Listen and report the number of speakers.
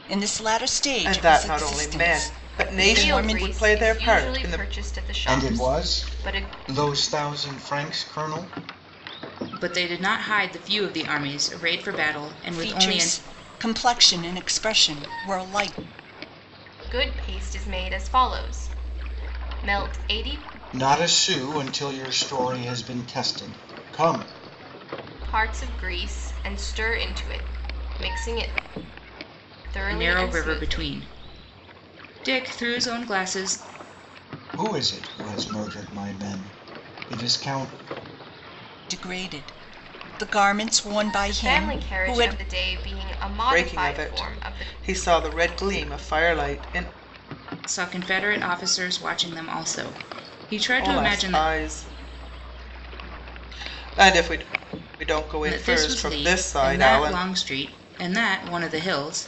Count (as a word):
five